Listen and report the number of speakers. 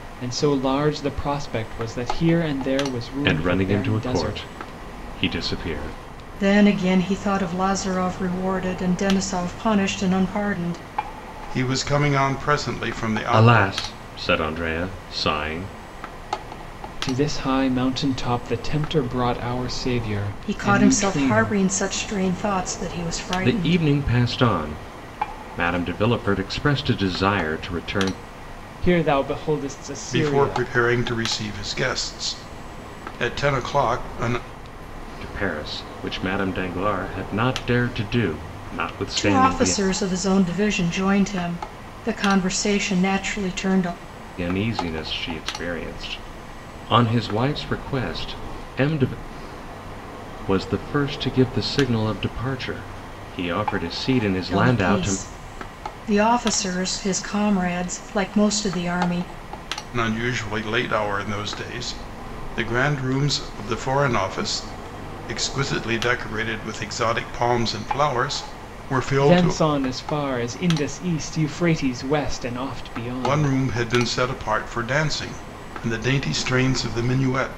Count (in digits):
4